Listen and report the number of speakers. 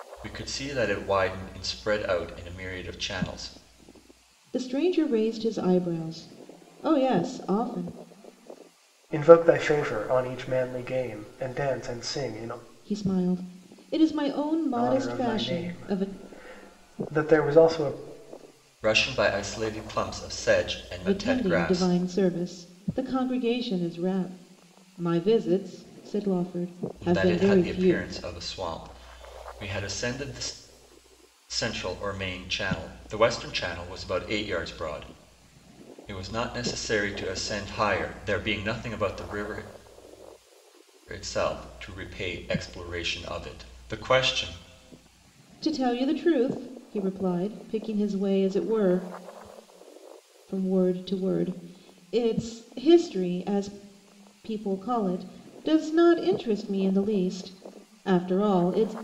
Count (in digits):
3